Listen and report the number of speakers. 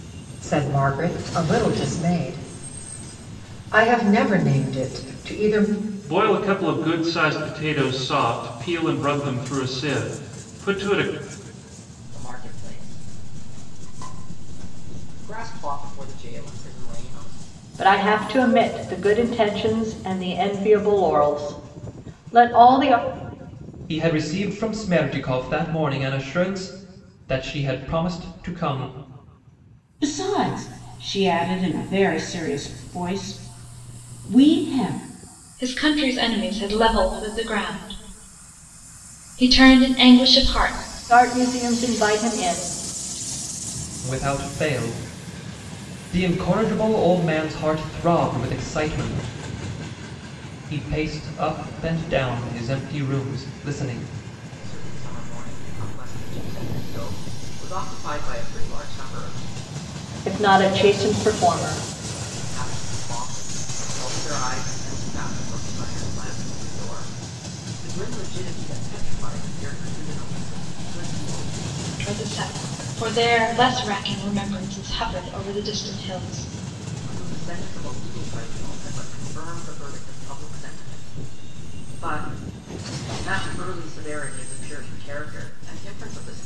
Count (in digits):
7